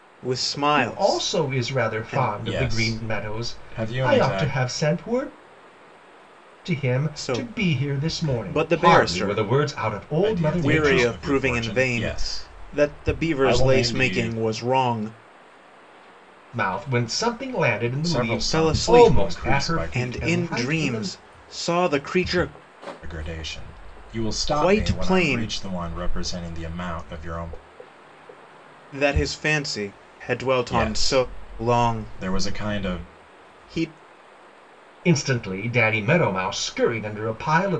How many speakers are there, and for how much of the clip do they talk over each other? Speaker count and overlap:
3, about 44%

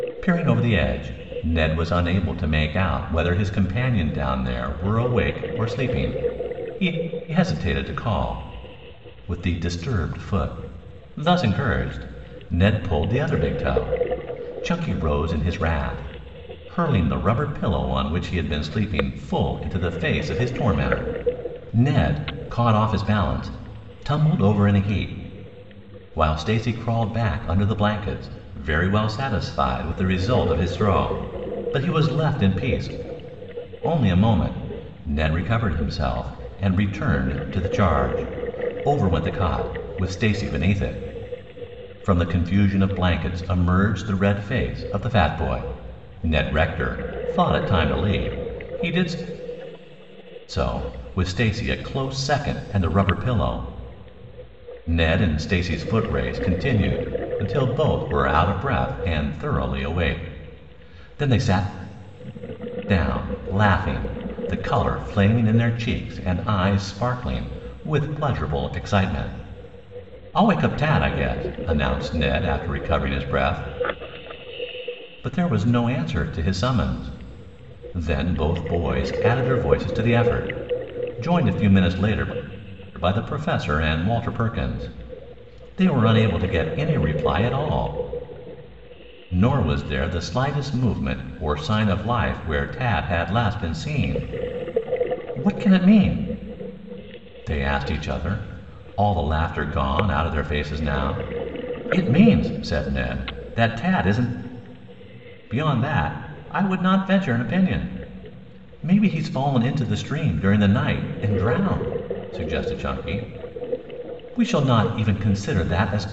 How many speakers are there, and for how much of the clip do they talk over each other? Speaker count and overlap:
1, no overlap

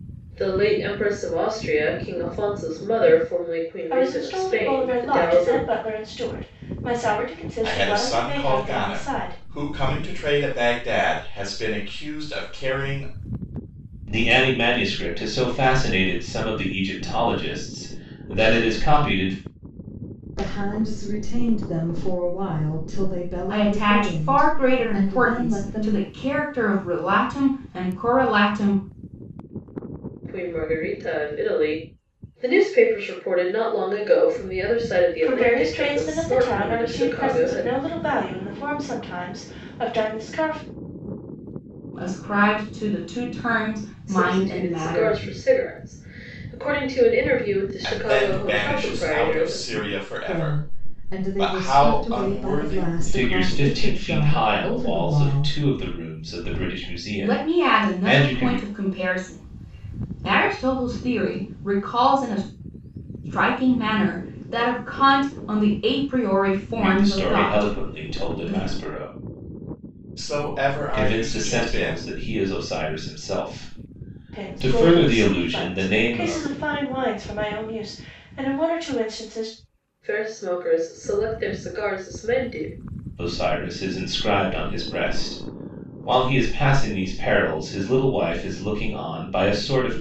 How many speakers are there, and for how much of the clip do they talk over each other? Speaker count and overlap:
6, about 26%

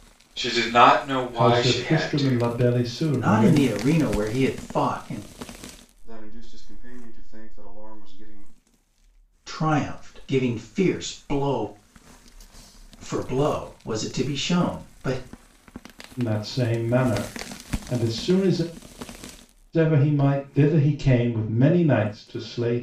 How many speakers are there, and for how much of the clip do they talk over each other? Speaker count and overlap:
4, about 7%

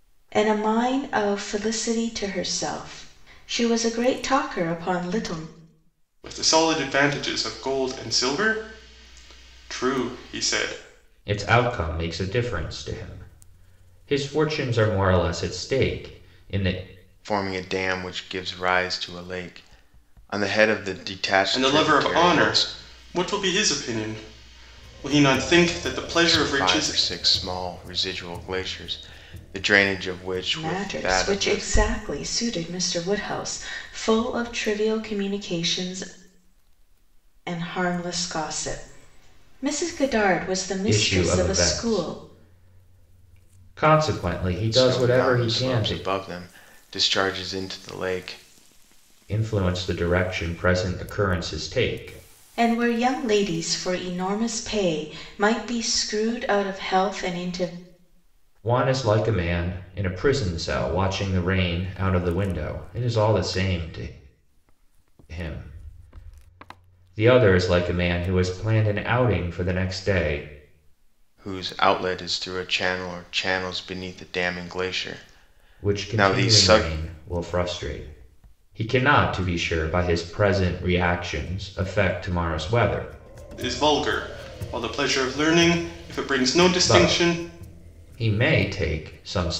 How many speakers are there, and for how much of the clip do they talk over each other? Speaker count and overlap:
4, about 8%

